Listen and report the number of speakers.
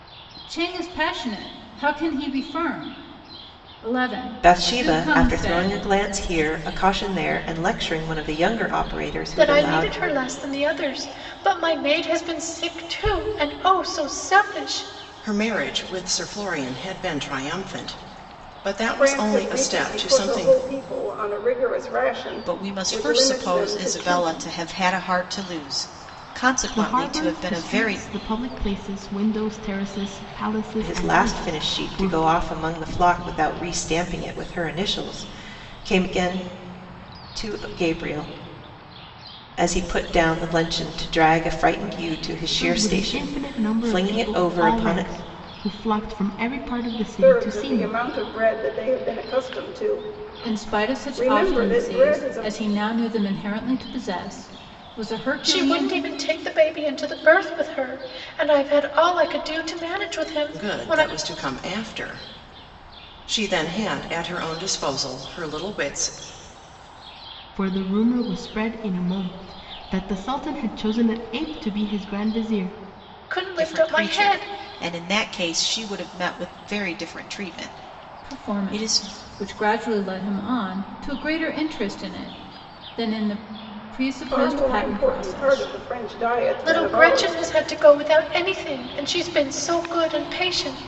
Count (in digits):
7